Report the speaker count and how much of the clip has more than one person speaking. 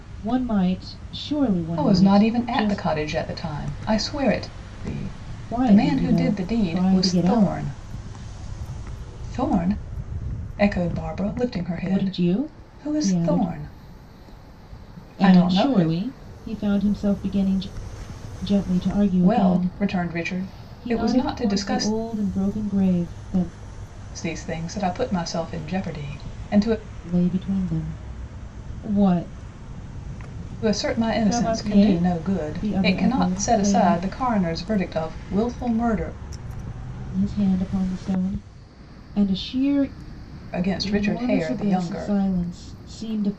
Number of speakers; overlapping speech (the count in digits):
2, about 27%